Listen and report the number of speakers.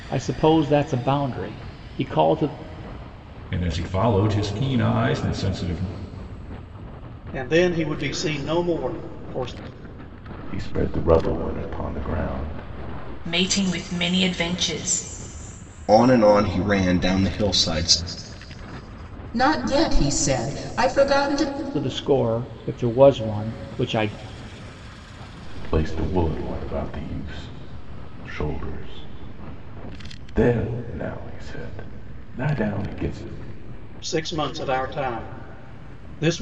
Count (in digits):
7